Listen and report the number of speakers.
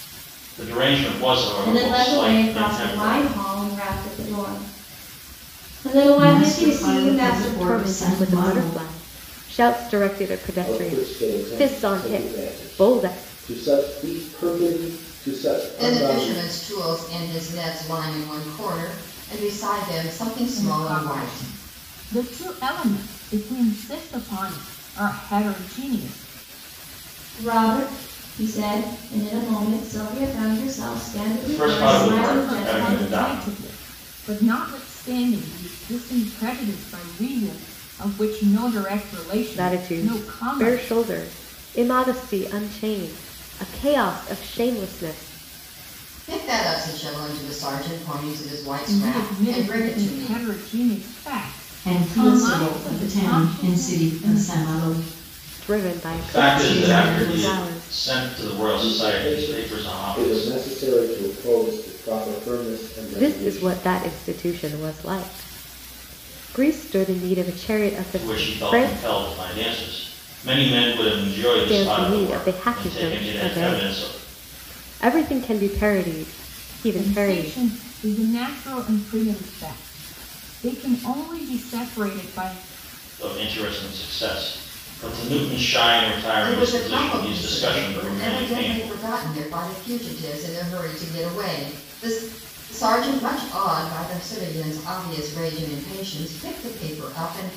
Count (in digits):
7